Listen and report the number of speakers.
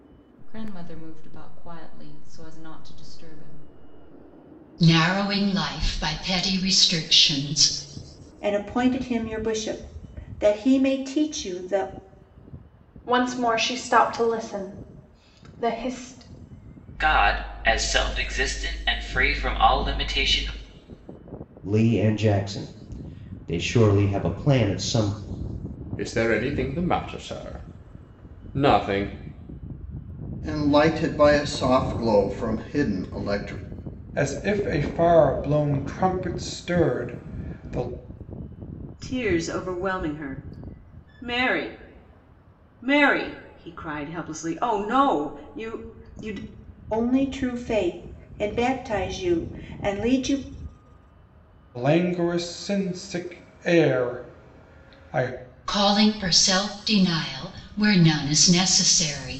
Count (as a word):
ten